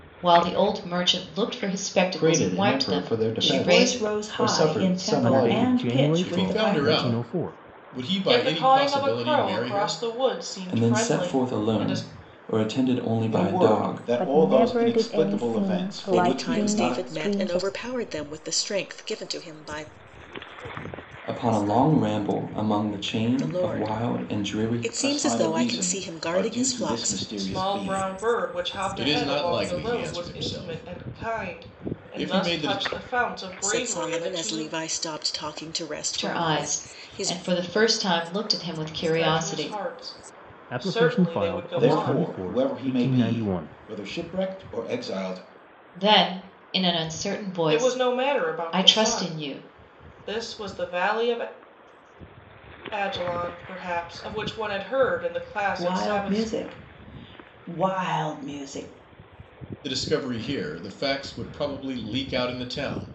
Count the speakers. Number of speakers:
ten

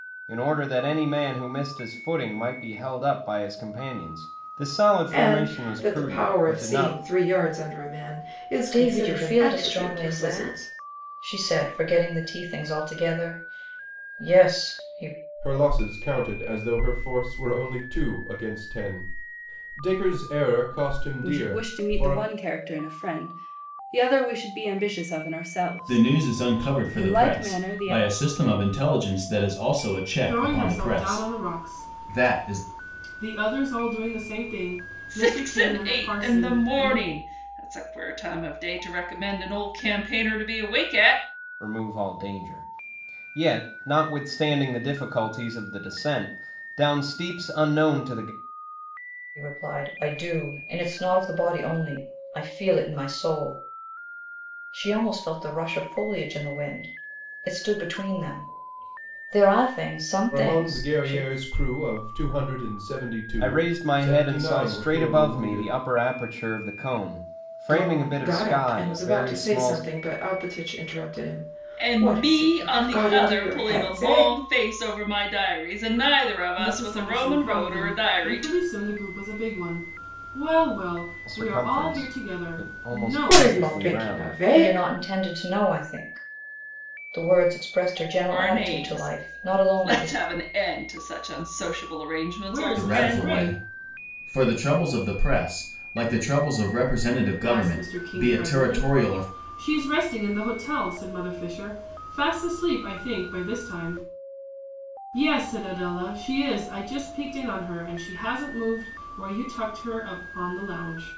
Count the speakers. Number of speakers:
eight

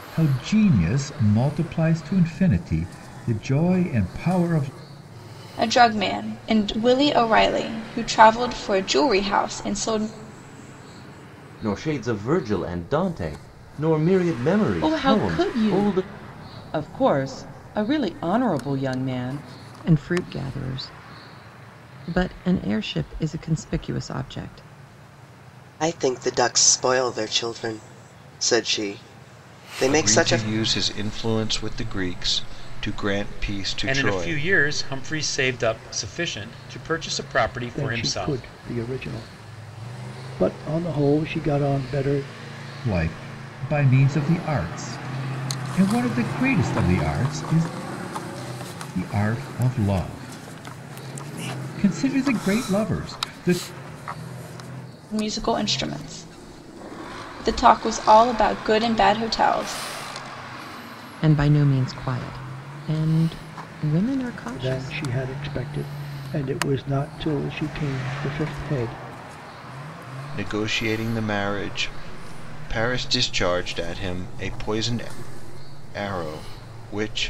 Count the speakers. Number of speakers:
nine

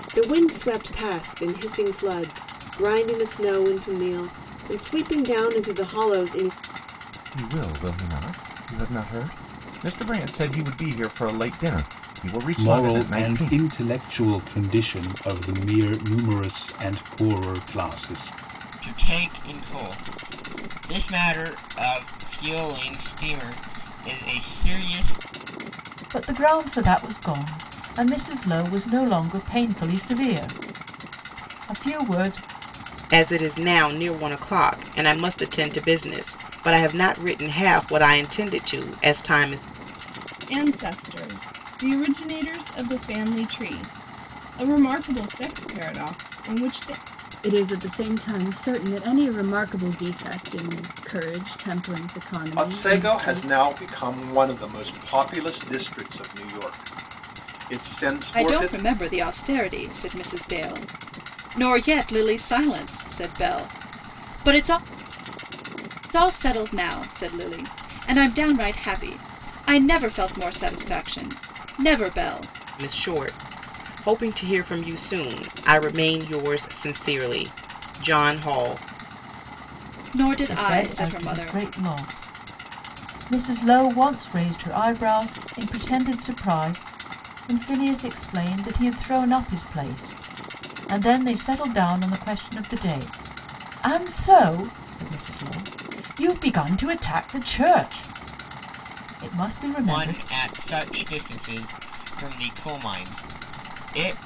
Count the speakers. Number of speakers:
ten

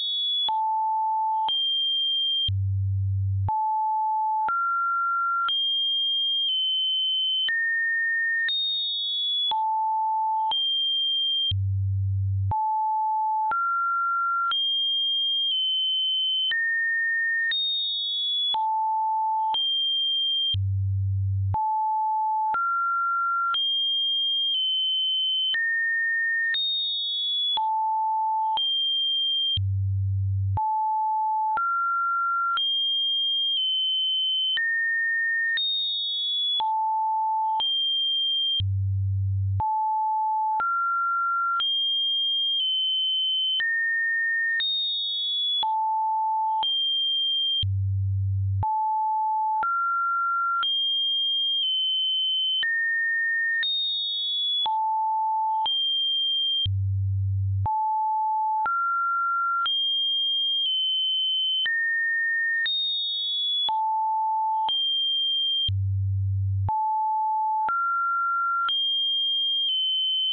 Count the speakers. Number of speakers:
zero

